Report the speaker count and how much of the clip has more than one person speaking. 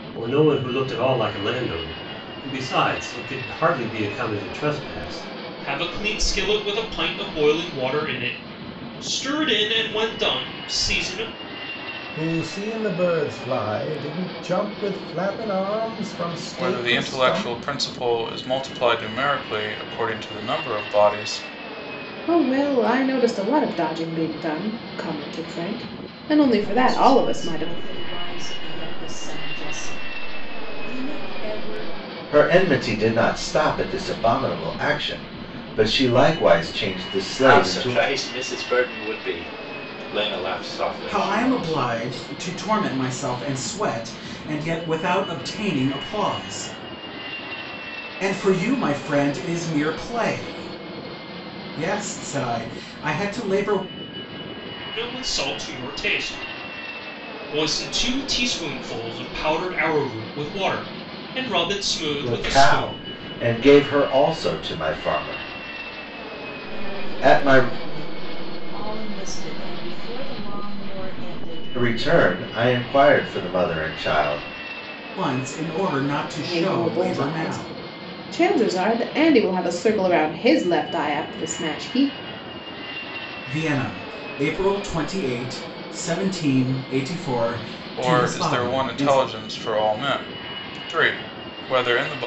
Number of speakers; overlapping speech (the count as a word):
nine, about 9%